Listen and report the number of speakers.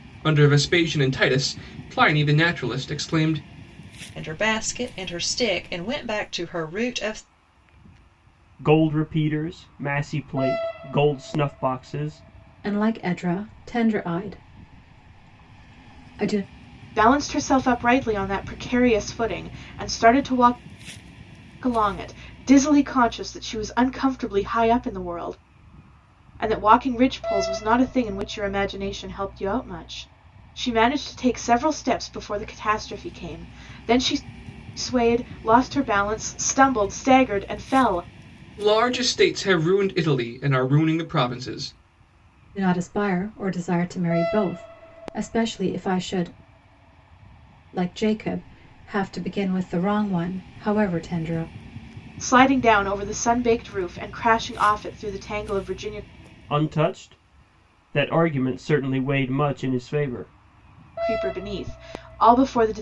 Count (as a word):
five